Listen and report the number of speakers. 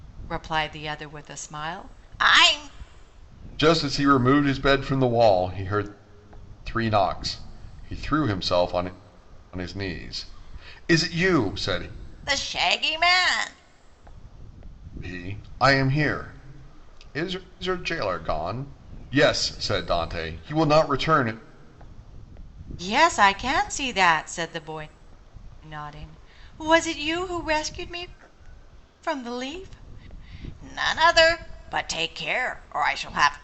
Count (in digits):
2